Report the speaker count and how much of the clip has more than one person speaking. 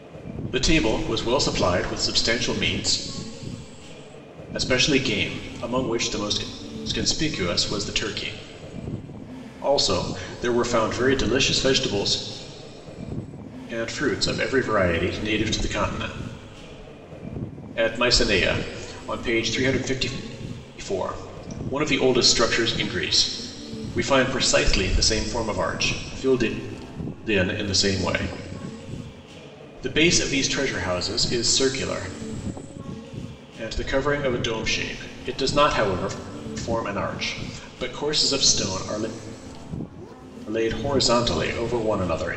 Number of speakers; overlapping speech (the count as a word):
one, no overlap